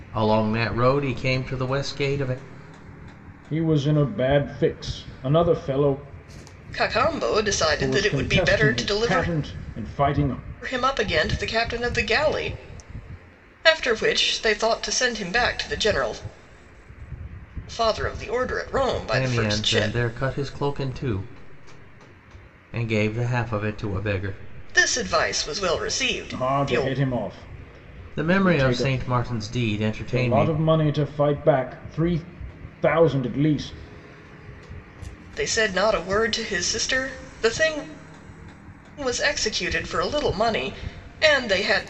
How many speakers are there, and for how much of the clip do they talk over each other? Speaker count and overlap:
3, about 10%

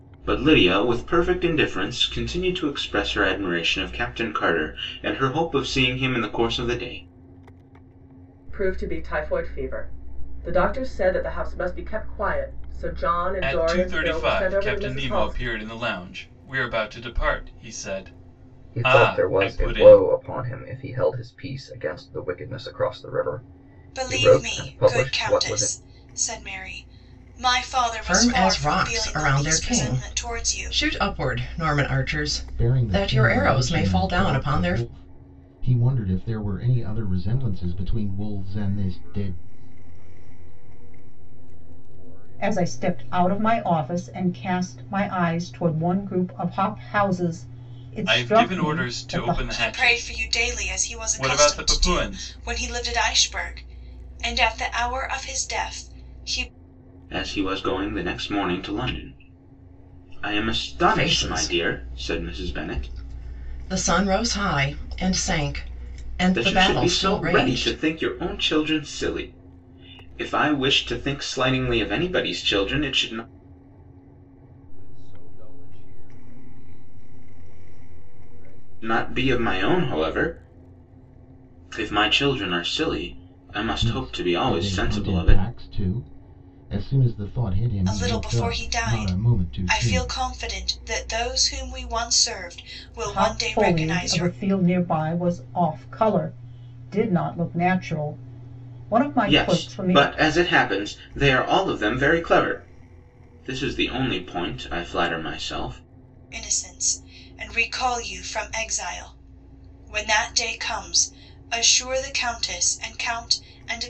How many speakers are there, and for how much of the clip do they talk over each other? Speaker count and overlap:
9, about 26%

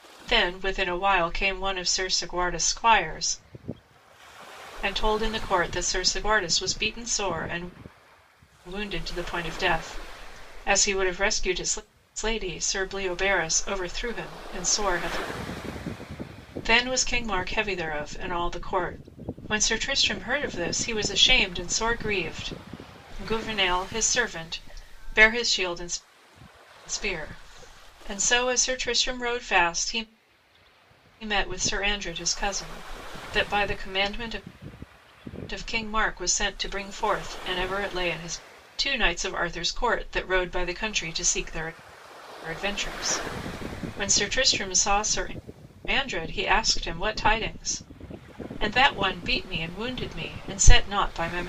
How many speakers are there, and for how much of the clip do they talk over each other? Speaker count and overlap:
1, no overlap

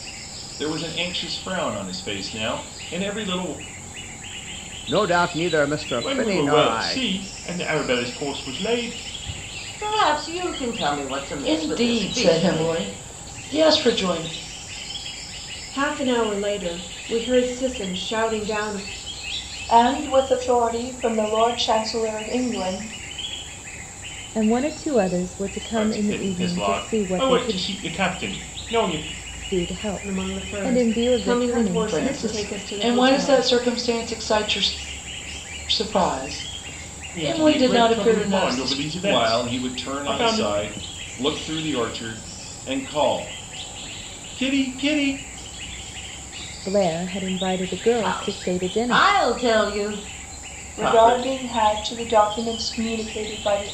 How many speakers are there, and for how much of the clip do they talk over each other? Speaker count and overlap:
8, about 23%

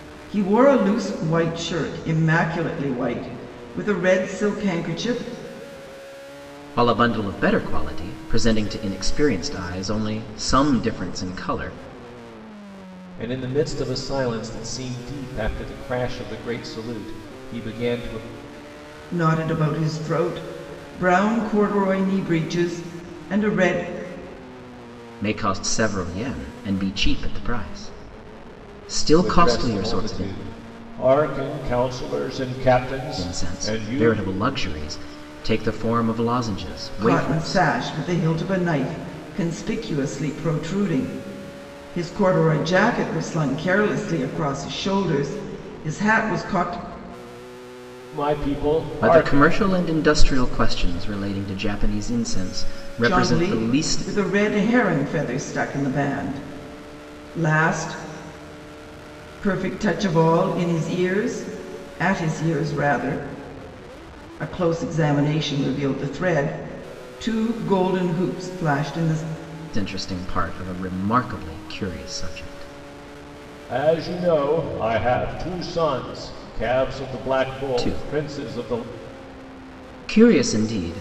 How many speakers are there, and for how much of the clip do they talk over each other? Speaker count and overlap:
3, about 7%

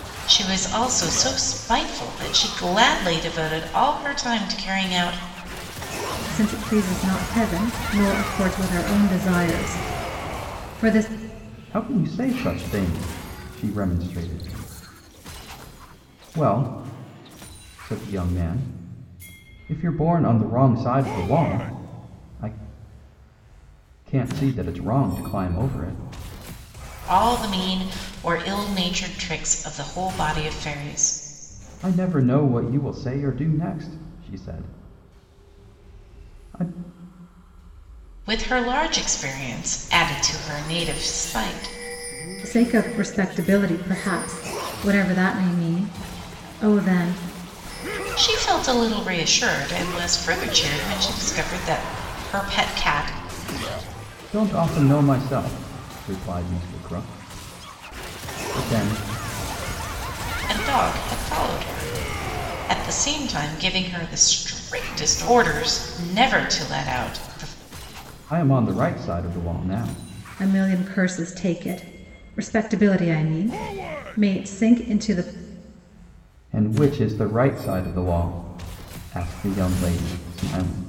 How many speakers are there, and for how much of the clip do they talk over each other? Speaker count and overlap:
3, no overlap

